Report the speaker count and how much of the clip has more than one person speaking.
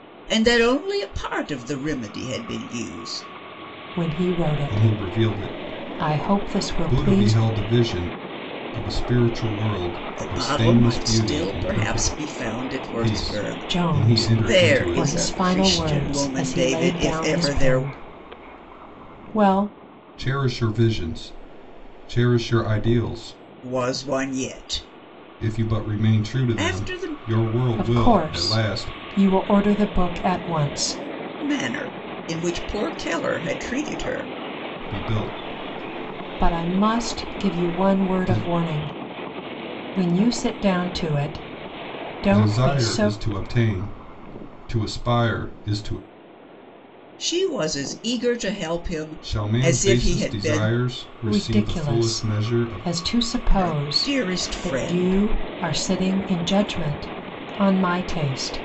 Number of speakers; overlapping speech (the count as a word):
three, about 35%